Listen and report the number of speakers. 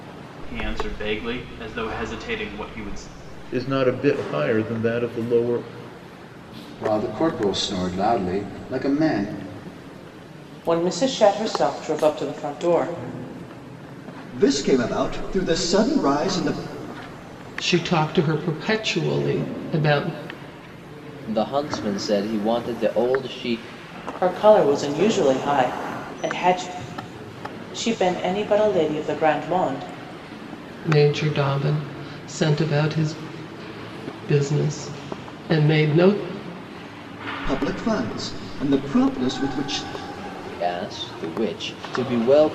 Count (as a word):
seven